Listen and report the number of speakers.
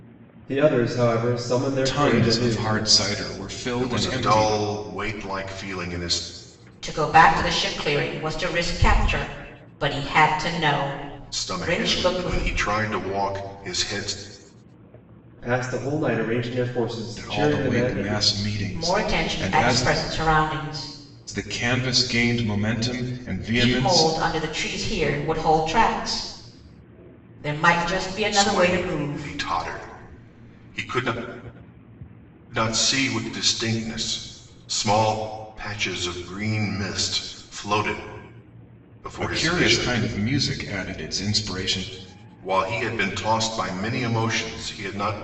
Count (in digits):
4